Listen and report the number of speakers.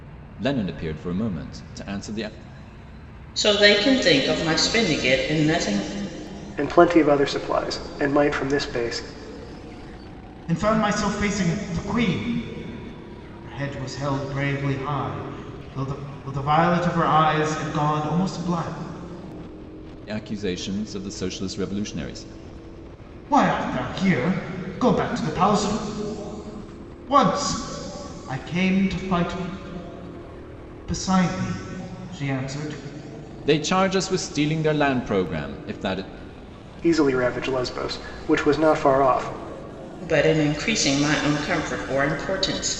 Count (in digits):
4